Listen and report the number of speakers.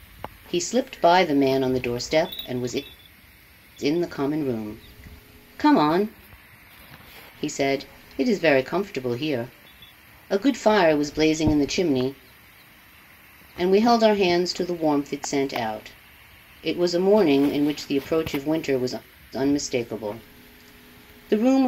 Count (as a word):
one